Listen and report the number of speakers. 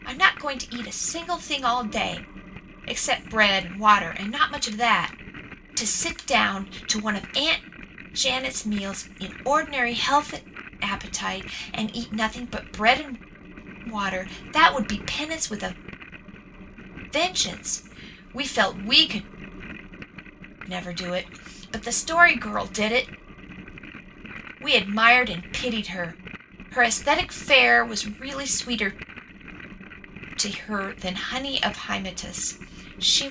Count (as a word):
one